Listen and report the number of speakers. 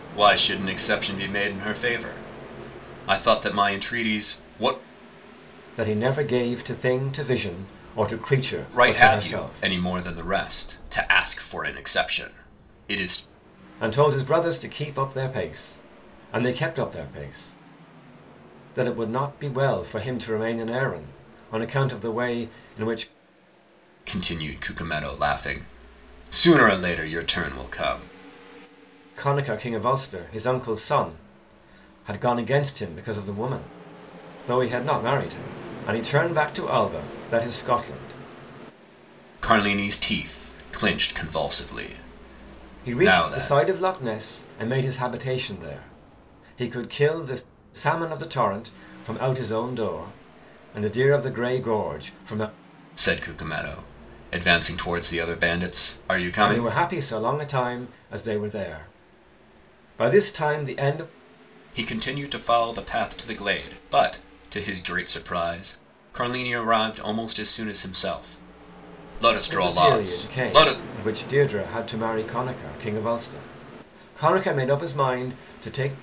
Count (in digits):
2